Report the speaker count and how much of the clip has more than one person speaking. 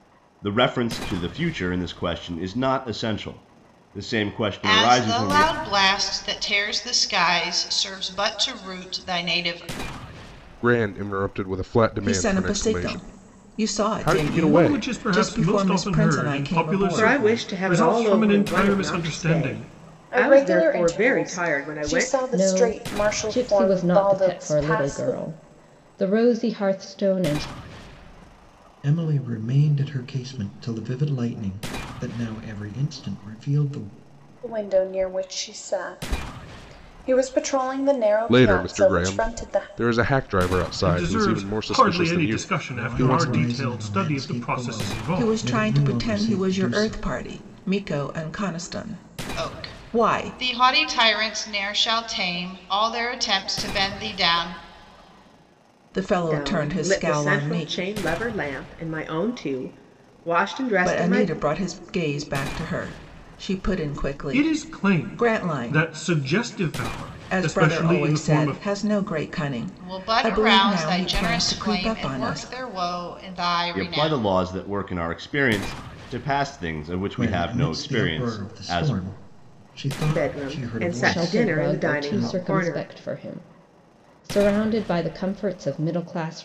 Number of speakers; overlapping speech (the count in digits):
9, about 41%